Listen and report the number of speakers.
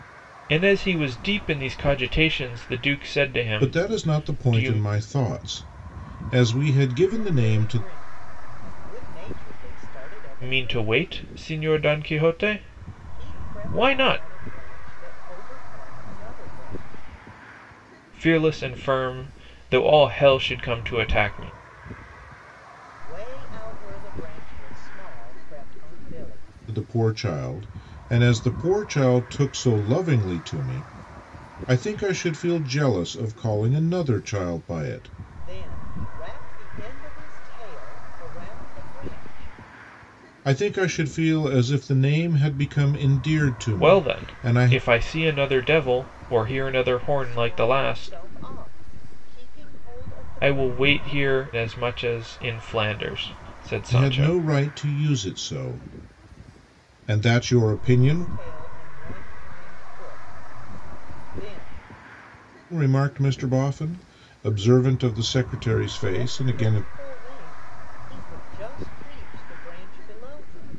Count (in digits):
3